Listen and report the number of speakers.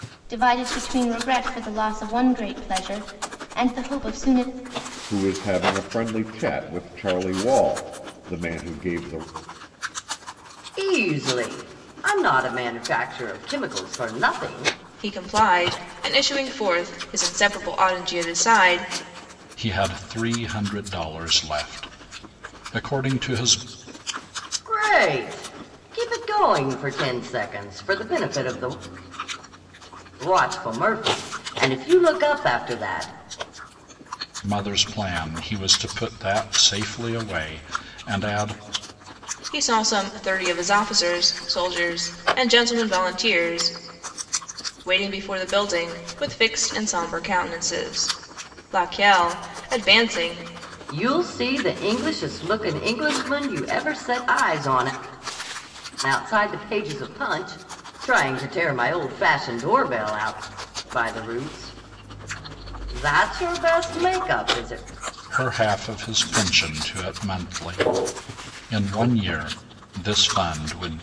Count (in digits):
5